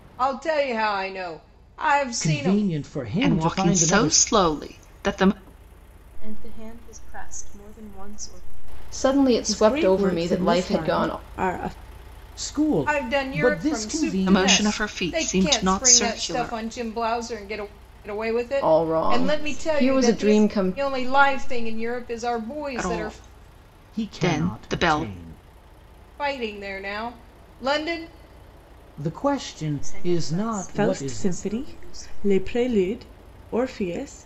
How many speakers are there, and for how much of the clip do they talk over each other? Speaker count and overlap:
six, about 41%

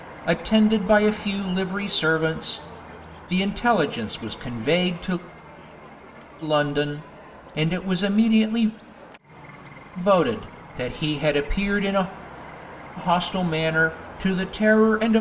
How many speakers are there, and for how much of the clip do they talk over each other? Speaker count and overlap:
one, no overlap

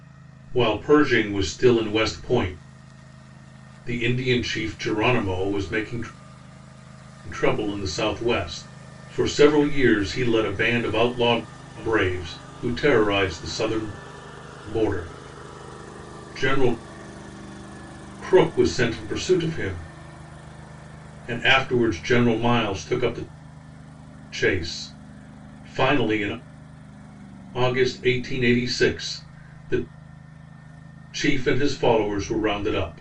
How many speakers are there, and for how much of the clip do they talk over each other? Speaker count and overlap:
one, no overlap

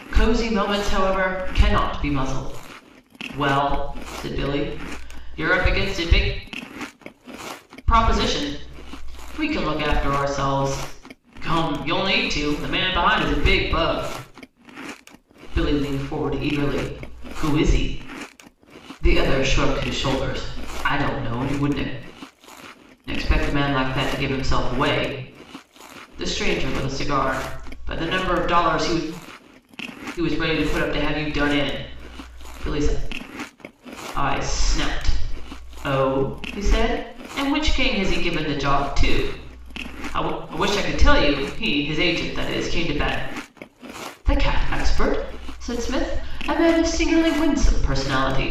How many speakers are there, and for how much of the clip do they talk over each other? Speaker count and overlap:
one, no overlap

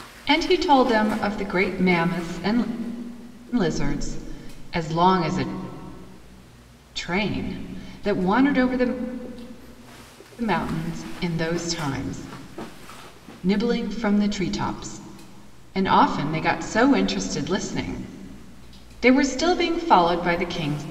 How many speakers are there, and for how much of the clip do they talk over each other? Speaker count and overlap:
one, no overlap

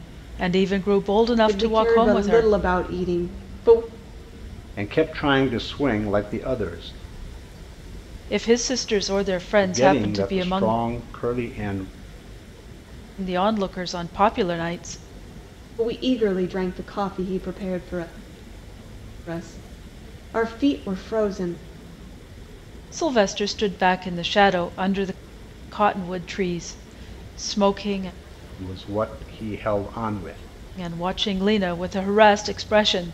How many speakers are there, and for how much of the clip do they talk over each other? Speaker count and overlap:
three, about 7%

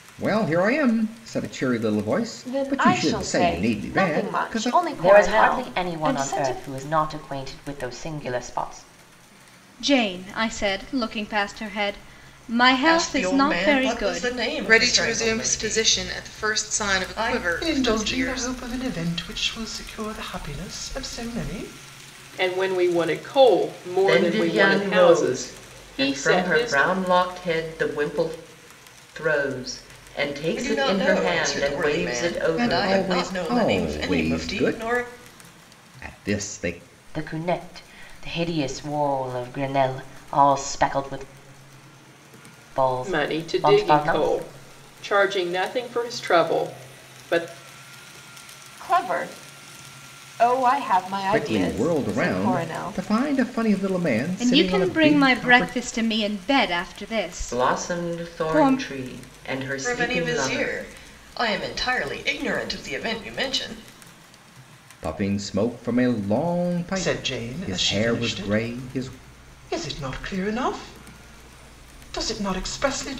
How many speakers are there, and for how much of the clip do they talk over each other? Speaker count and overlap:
nine, about 35%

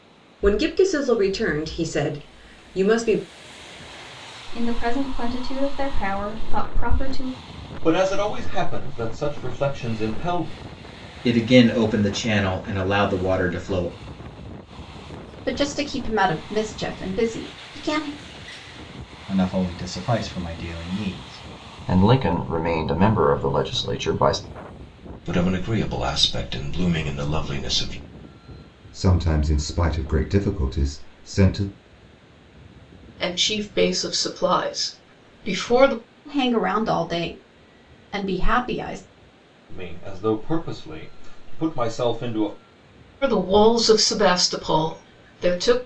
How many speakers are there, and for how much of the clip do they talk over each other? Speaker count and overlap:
ten, no overlap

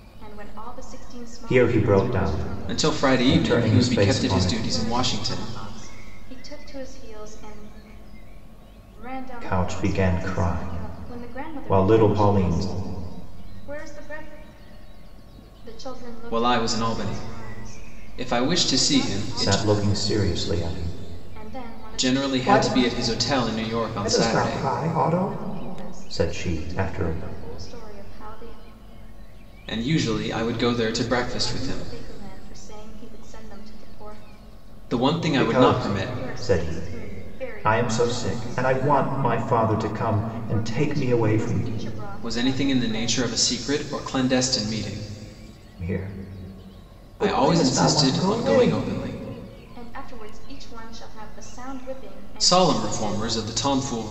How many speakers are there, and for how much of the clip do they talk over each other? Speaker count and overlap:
three, about 48%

